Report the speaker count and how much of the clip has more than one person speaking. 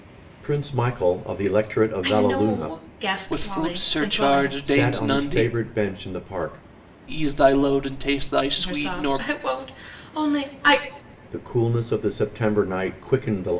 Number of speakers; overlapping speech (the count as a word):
three, about 26%